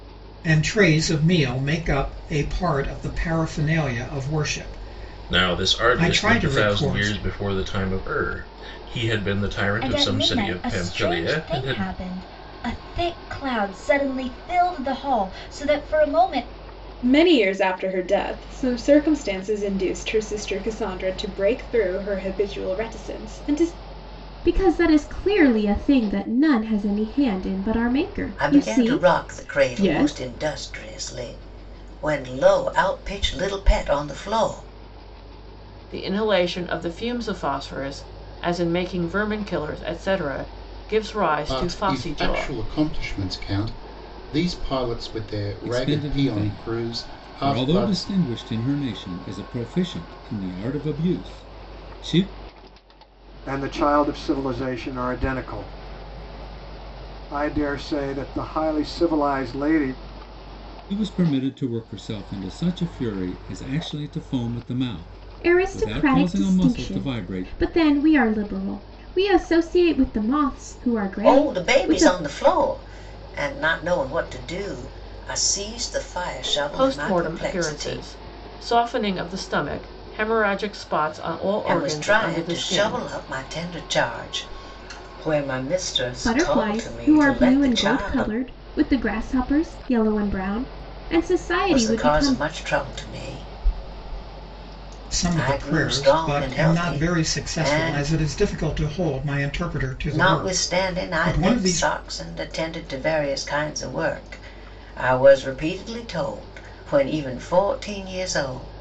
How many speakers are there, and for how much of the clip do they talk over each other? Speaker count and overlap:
10, about 21%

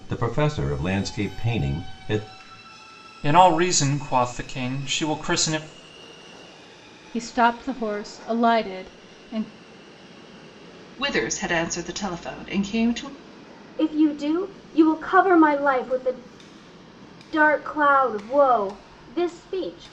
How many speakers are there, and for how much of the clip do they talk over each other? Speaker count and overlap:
5, no overlap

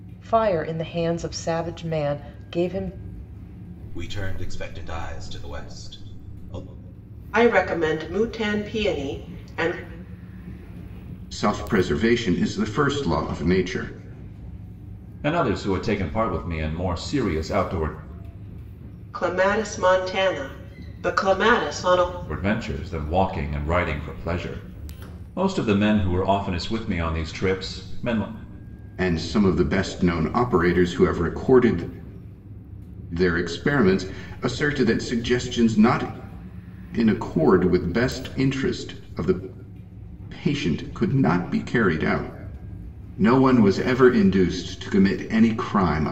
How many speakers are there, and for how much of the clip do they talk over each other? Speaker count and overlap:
5, no overlap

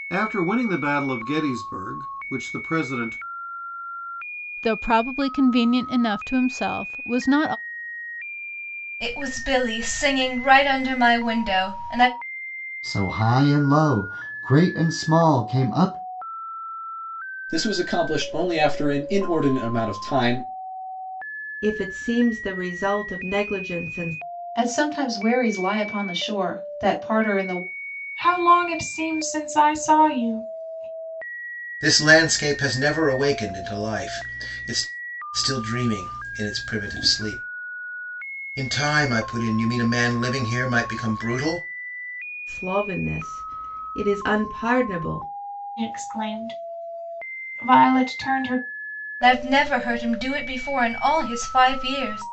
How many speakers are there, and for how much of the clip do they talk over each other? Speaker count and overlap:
9, no overlap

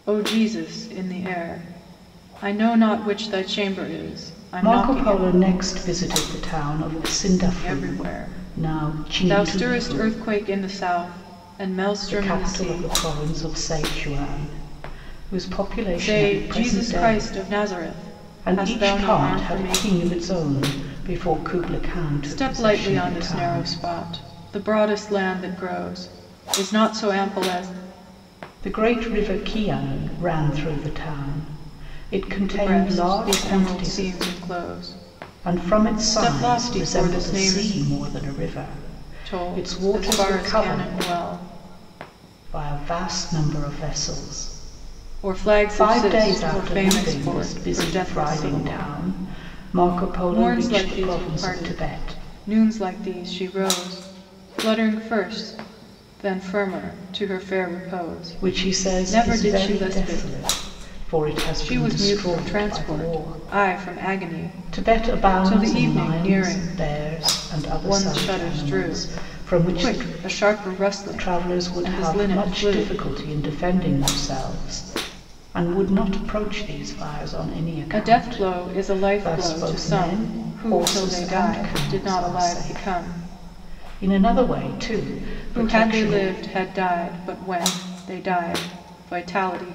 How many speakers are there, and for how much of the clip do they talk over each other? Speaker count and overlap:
2, about 39%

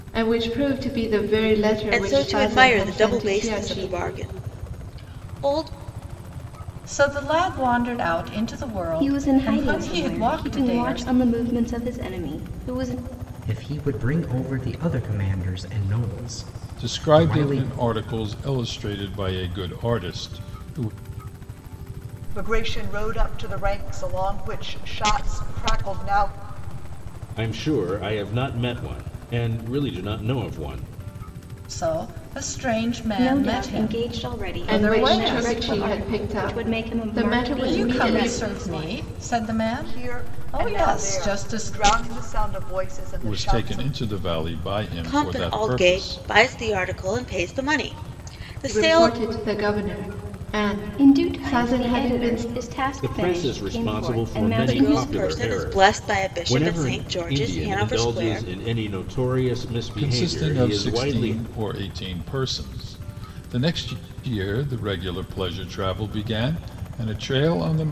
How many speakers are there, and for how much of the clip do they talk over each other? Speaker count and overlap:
8, about 35%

